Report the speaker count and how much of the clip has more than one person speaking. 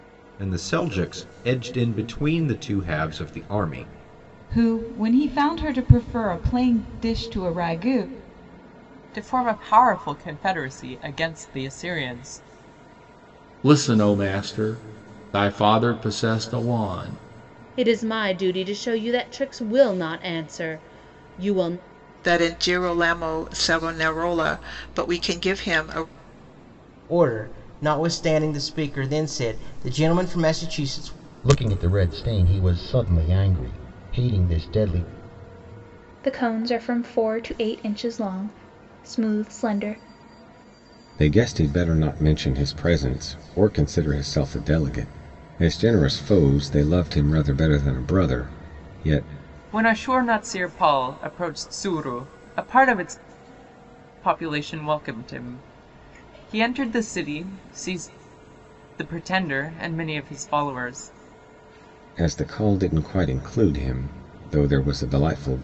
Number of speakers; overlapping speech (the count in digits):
10, no overlap